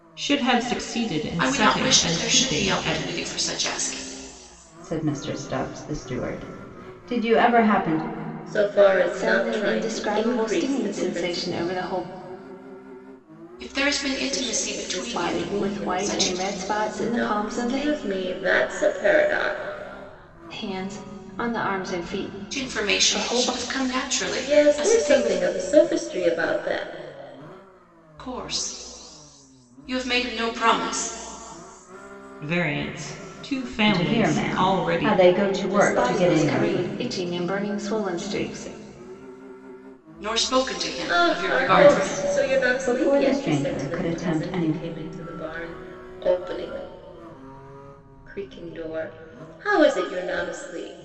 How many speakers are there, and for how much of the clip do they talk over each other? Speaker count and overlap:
five, about 32%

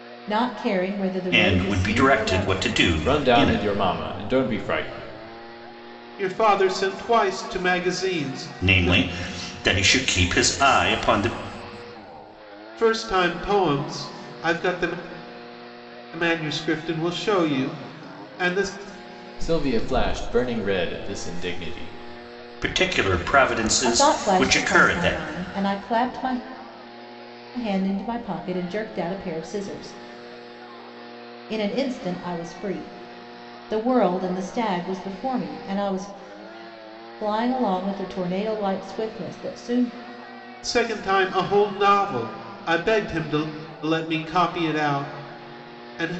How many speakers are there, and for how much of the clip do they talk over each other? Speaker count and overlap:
four, about 9%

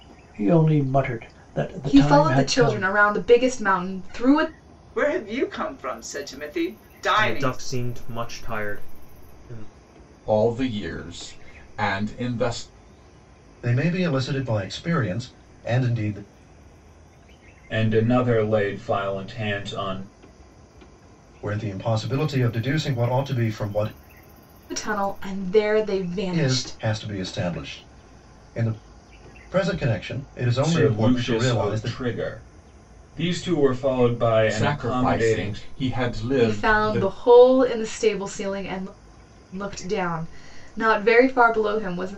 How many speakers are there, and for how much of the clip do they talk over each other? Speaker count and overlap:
seven, about 13%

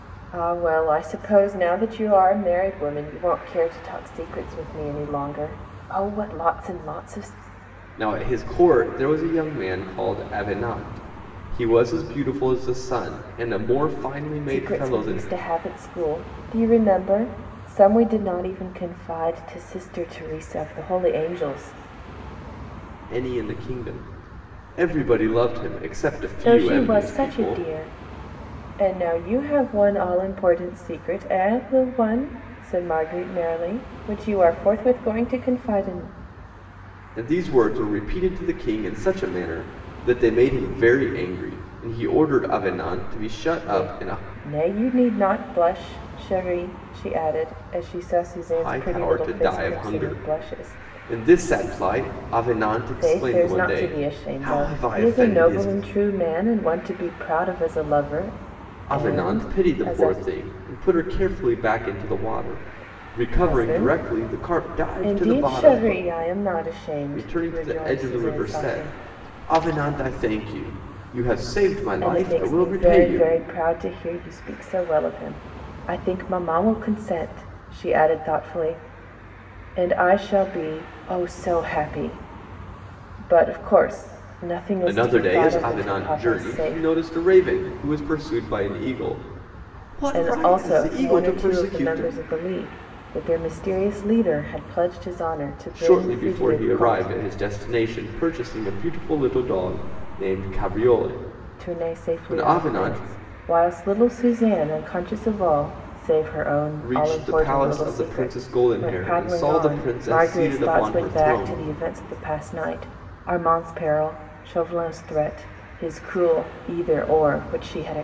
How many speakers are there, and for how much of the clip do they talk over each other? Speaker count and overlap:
two, about 23%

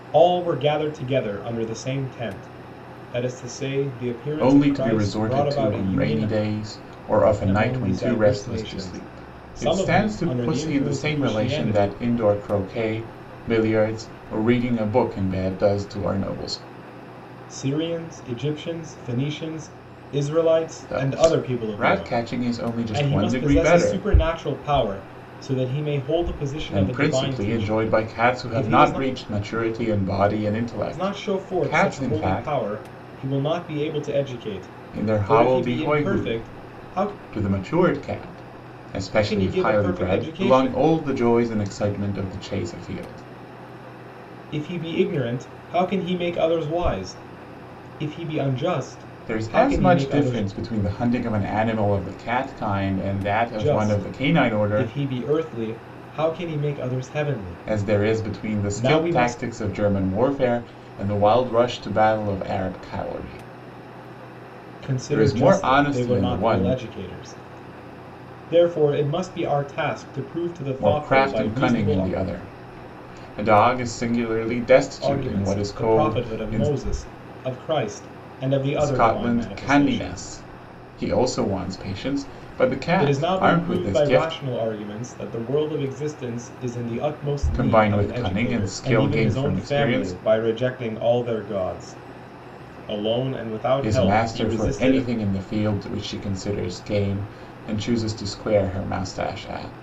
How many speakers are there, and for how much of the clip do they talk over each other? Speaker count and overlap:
two, about 33%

